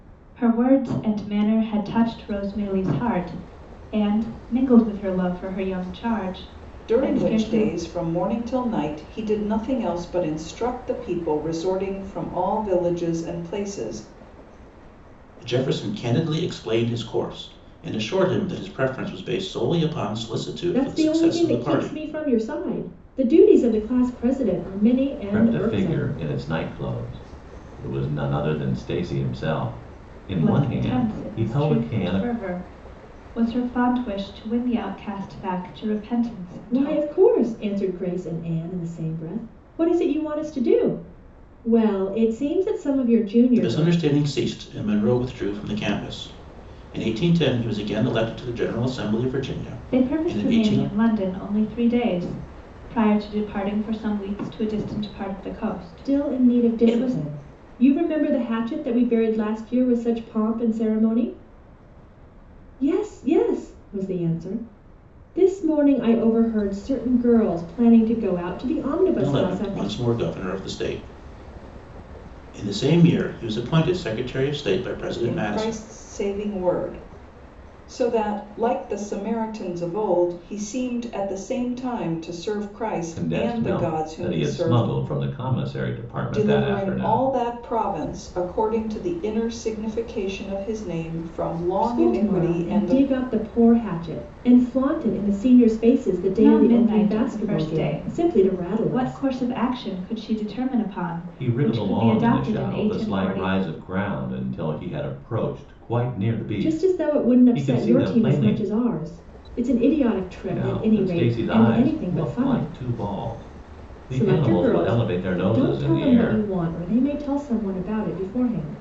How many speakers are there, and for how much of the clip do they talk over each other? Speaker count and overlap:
5, about 22%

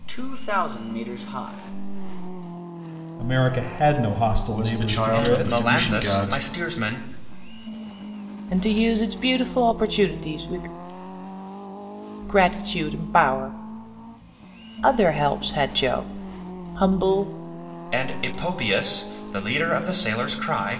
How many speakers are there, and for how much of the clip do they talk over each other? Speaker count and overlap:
5, about 10%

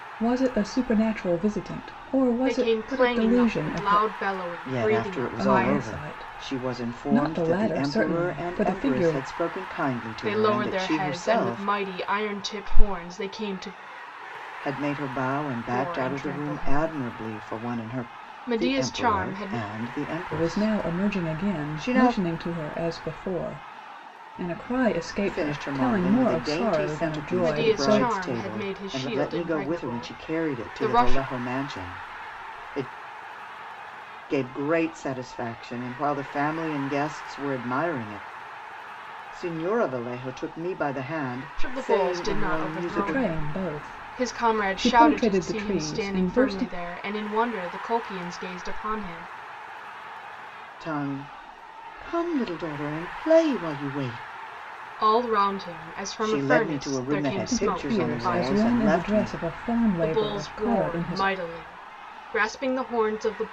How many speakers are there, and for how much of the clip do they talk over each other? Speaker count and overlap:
3, about 46%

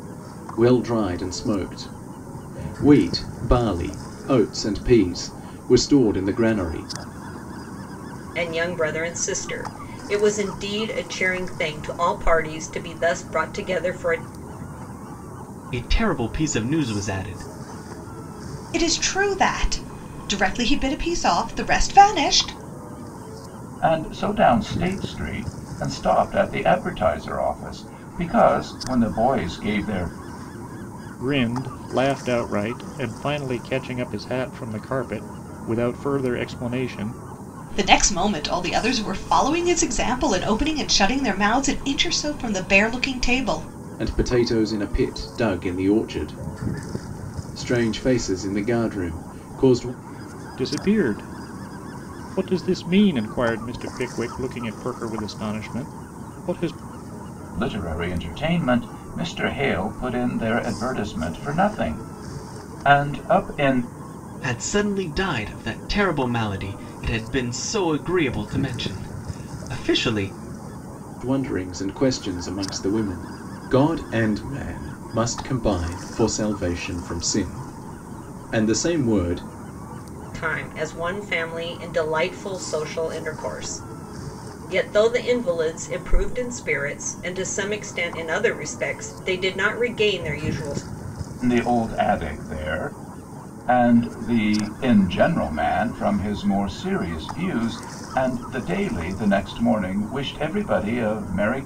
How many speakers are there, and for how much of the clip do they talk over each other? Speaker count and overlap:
6, no overlap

